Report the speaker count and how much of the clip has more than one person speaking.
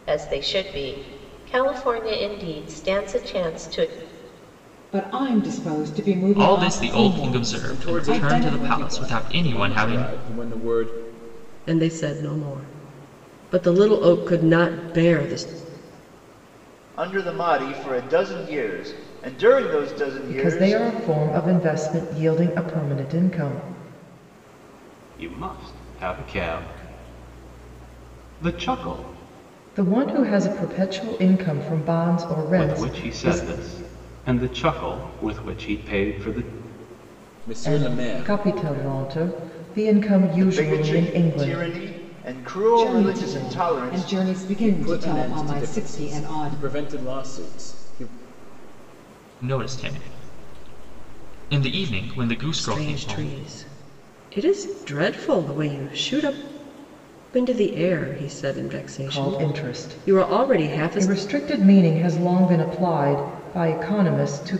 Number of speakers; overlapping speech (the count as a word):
eight, about 21%